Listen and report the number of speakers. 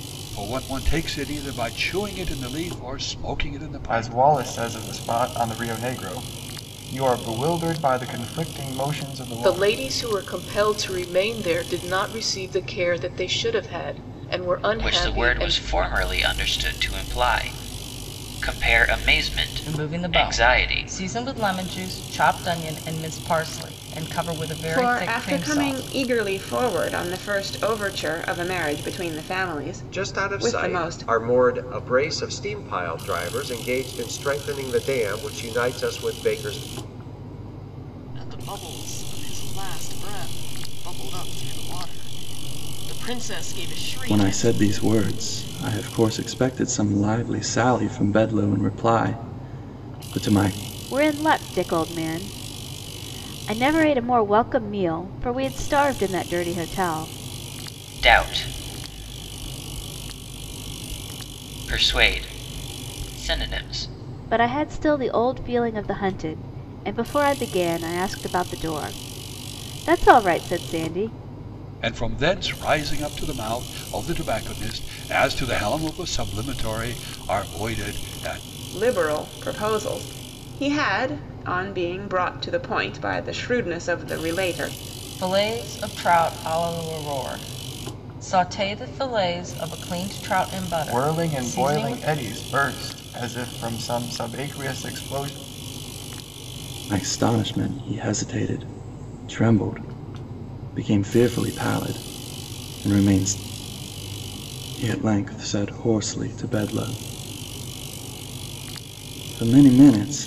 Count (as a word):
ten